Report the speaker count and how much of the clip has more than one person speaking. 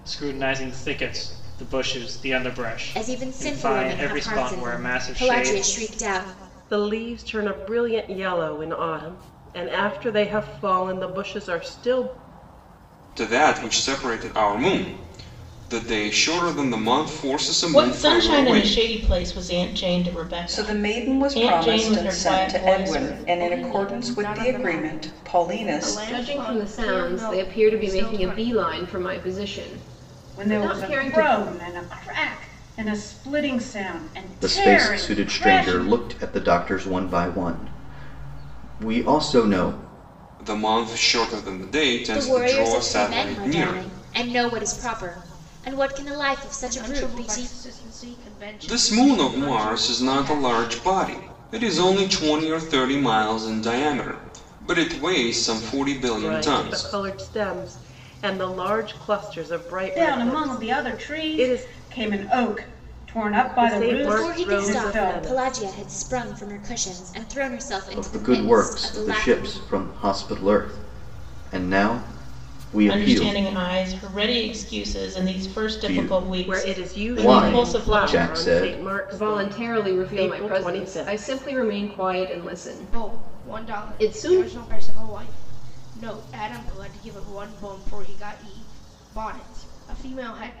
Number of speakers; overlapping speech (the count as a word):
ten, about 36%